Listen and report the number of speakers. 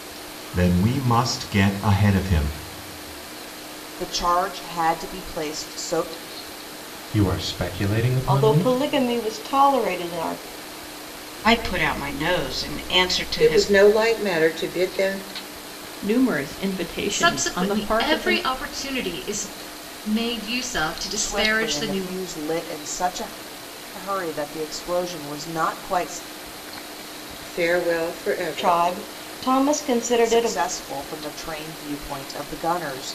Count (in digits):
8